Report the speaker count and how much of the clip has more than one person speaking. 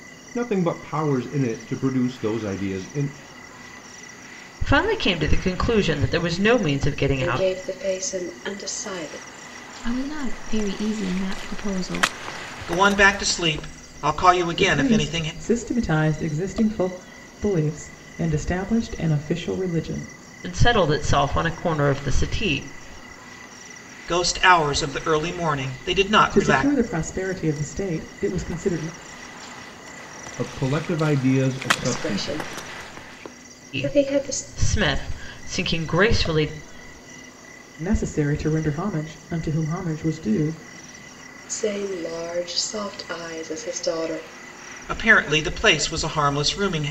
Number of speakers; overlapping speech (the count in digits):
6, about 7%